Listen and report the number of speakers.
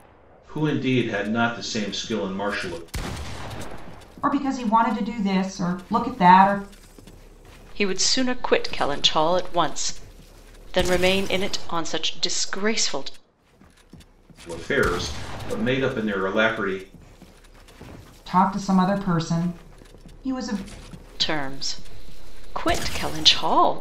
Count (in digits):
3